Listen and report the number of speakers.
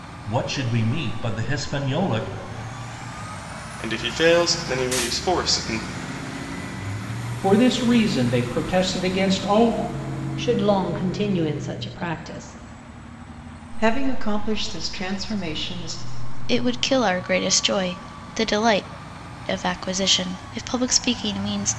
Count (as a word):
six